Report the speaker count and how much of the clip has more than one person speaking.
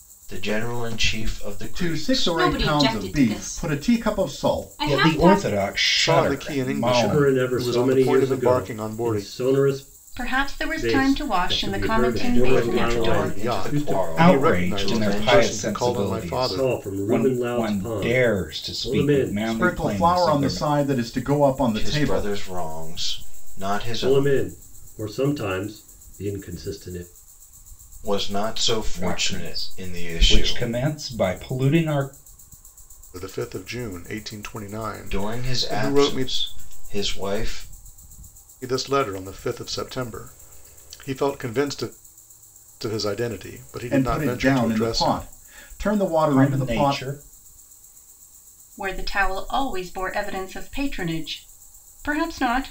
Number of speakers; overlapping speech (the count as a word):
seven, about 44%